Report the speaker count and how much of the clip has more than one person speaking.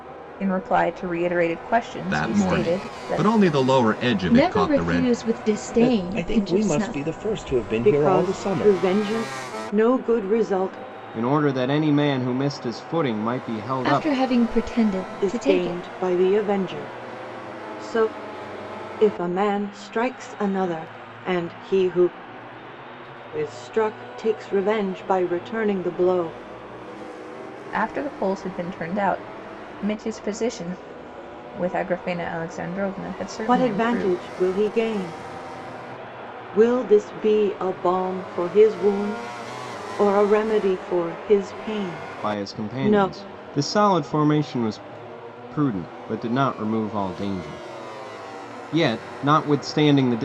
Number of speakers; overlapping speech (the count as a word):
six, about 15%